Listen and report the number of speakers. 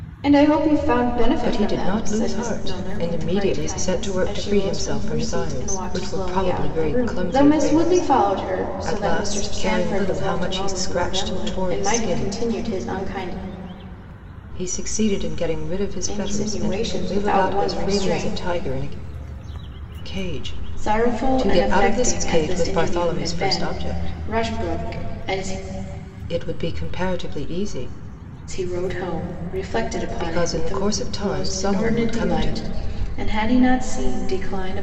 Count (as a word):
two